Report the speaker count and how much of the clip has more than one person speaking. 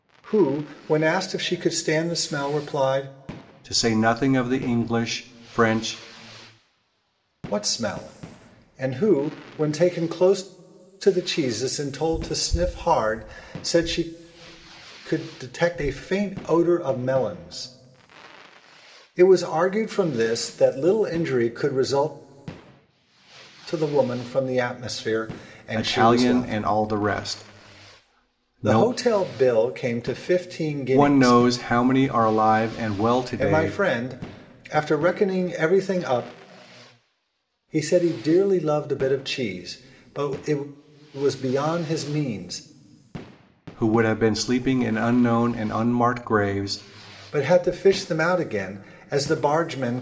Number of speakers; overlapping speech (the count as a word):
two, about 4%